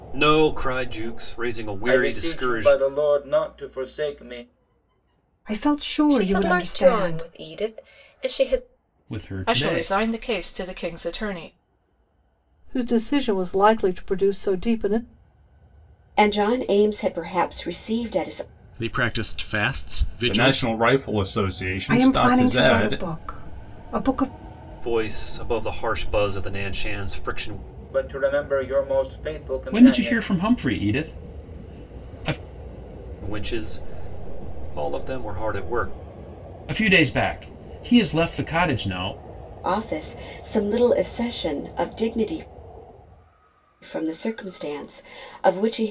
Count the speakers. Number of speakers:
10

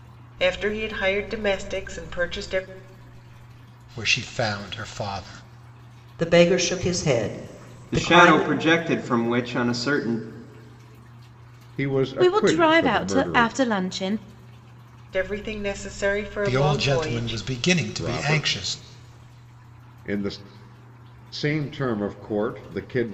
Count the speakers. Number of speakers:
6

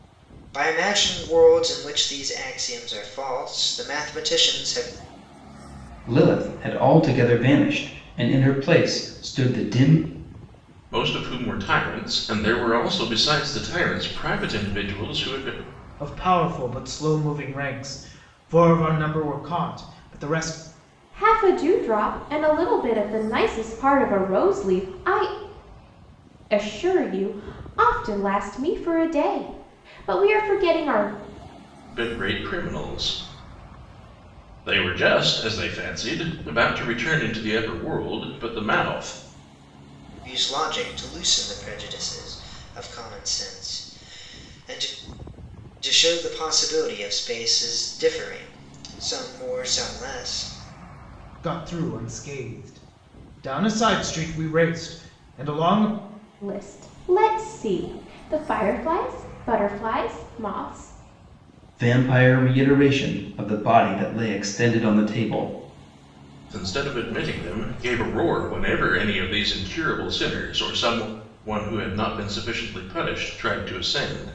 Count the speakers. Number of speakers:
5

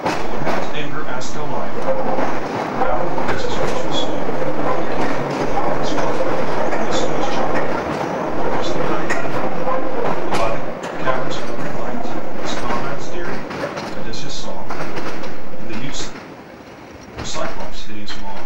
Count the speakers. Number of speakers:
1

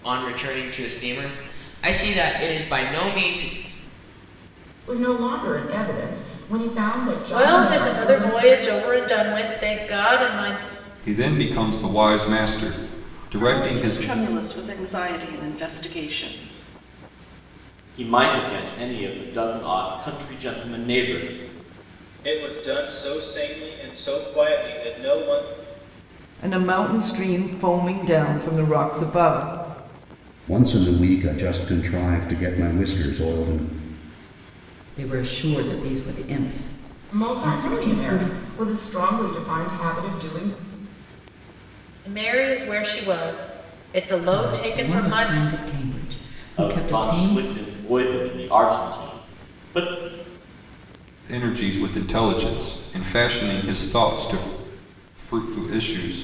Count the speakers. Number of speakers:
10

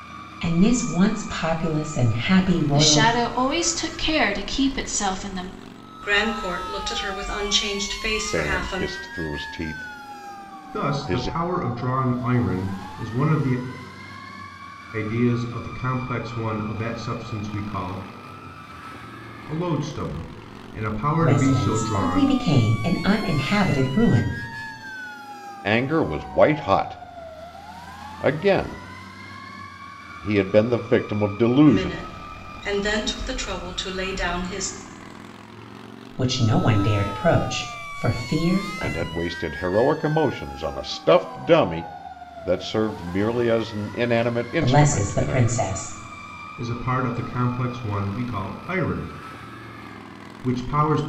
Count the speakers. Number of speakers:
5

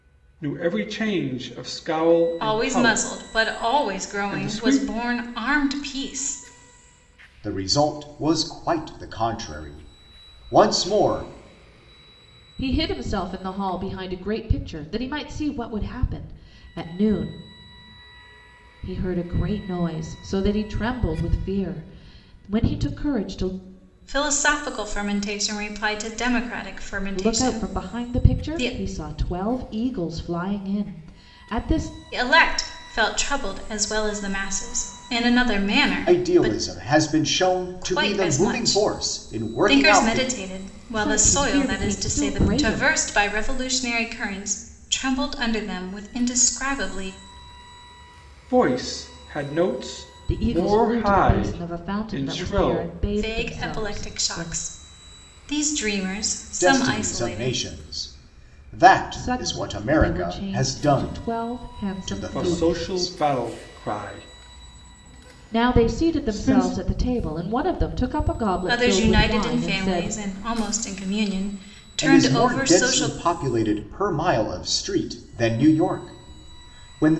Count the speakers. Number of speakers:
4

